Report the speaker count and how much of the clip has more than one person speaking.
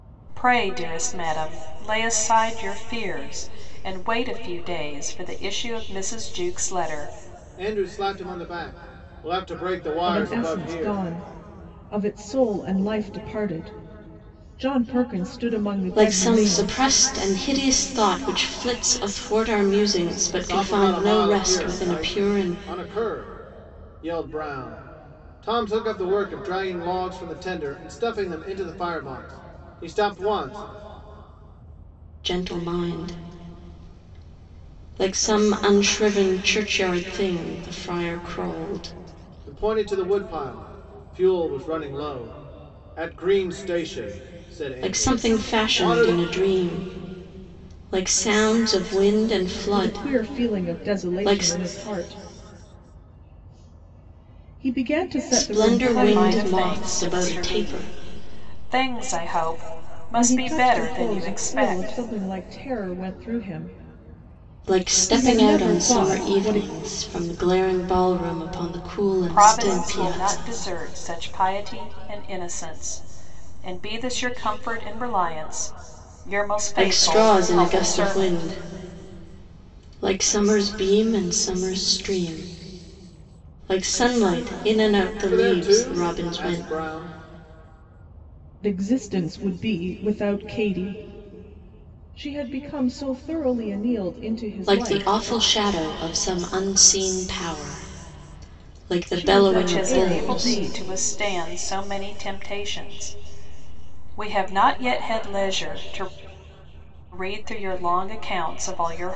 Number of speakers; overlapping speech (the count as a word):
four, about 20%